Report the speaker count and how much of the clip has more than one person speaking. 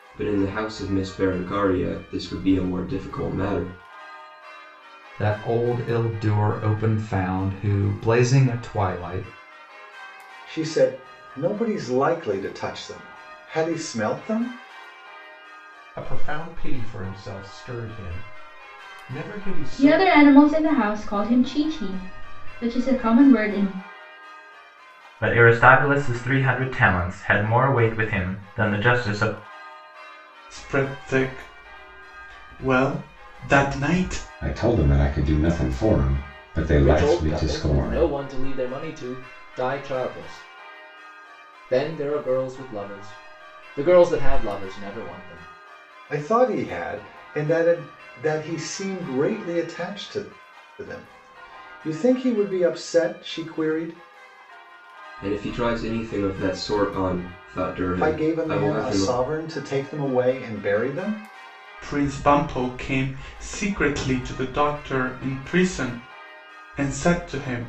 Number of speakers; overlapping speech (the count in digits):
9, about 4%